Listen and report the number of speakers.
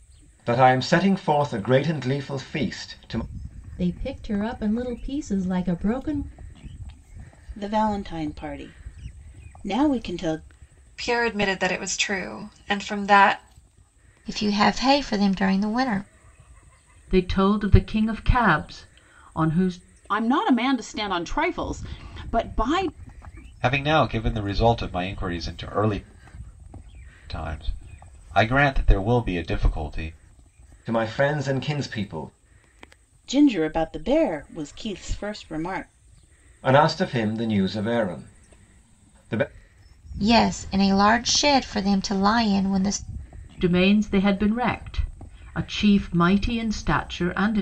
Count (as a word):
eight